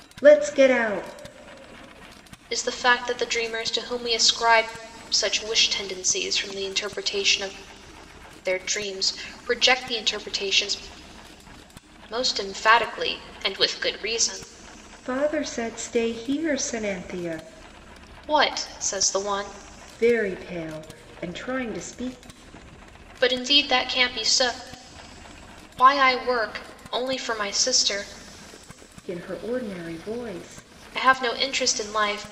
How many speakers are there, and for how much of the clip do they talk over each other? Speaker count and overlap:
2, no overlap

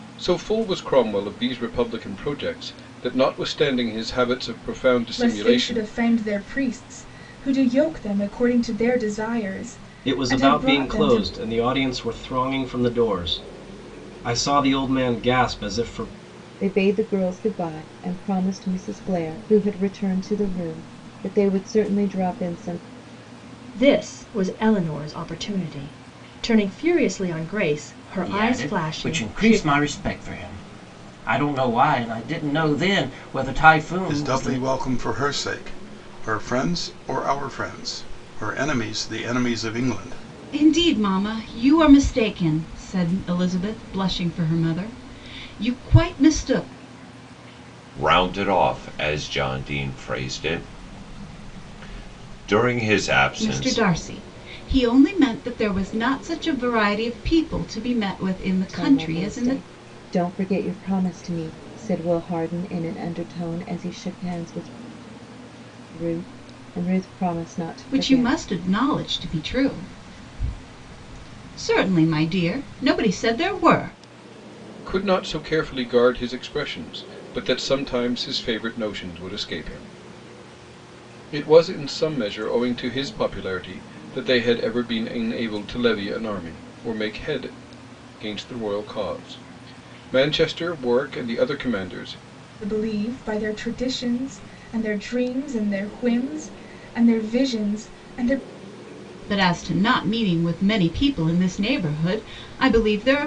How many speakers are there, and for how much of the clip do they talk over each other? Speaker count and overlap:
9, about 6%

